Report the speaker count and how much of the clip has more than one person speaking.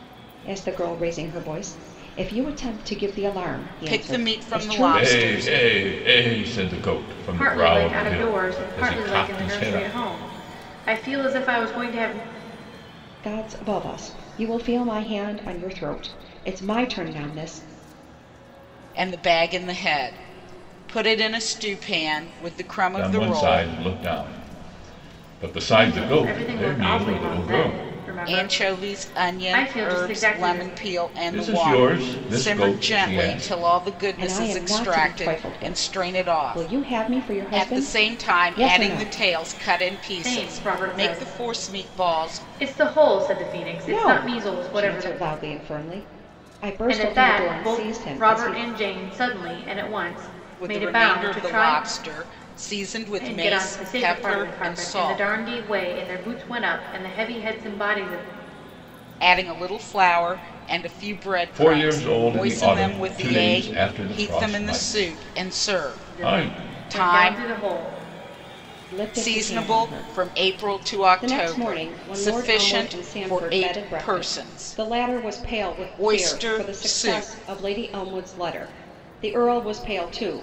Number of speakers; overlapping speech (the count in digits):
4, about 47%